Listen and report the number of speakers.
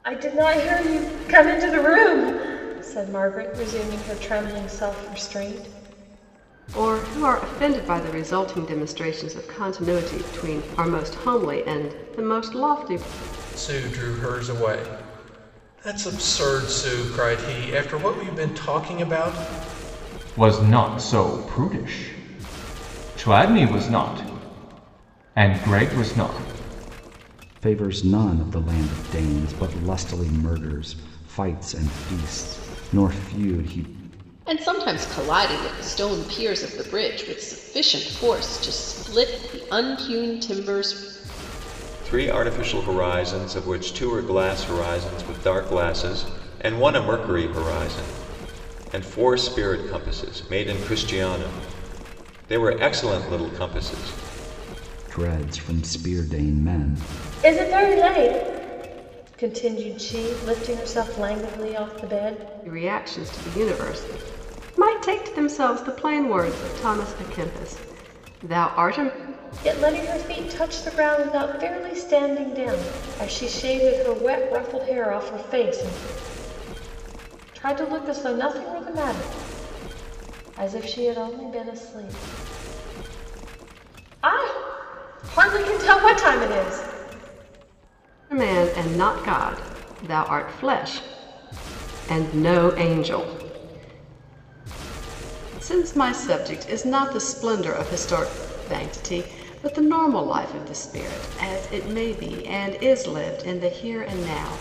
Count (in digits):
7